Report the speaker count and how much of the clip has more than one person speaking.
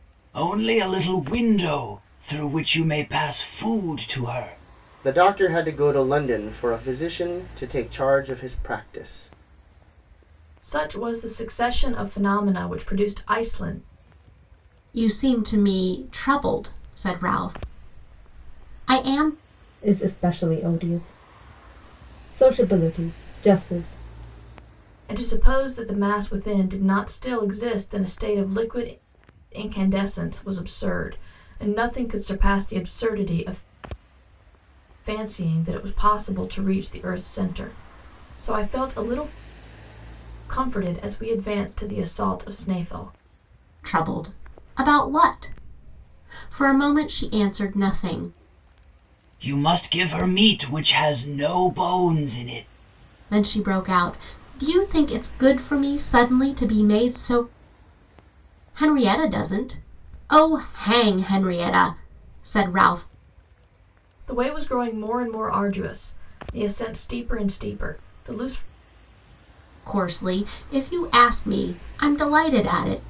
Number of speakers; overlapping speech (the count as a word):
five, no overlap